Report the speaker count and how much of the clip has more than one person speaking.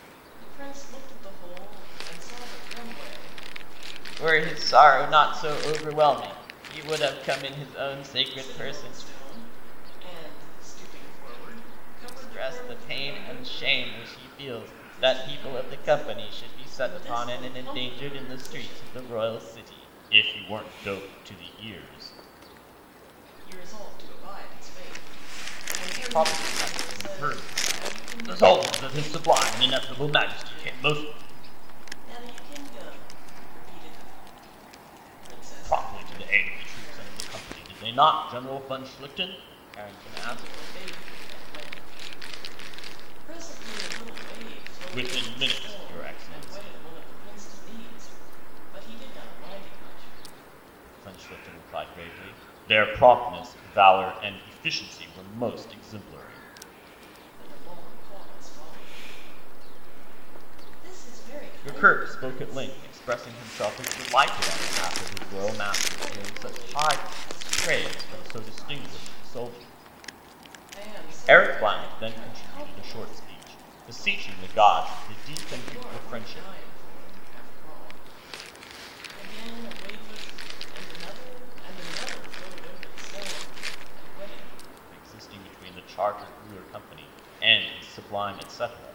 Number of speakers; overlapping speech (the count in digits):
2, about 32%